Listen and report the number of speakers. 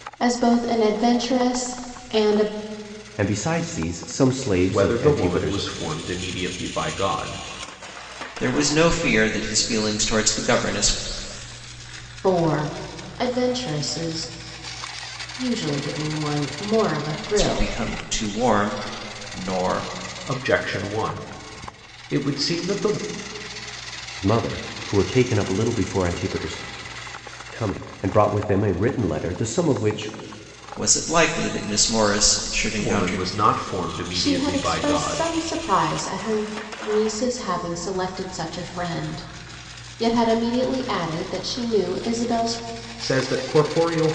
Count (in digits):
4